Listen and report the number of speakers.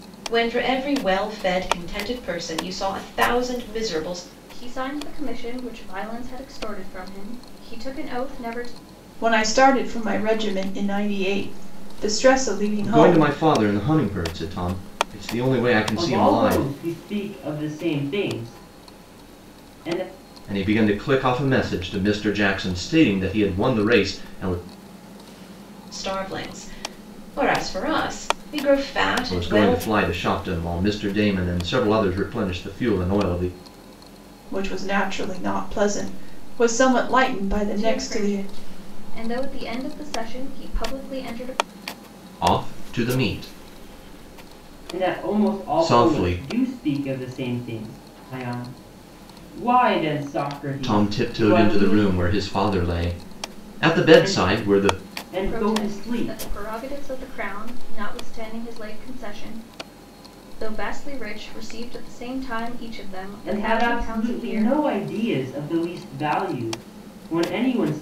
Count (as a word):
five